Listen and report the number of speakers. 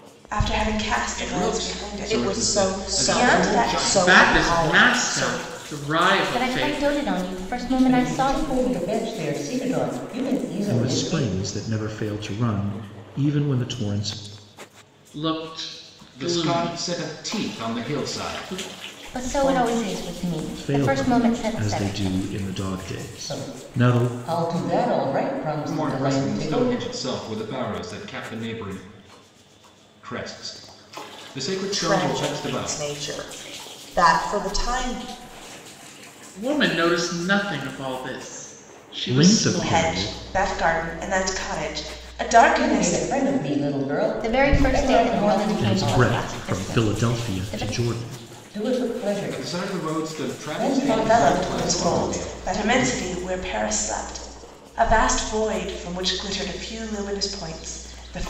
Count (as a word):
seven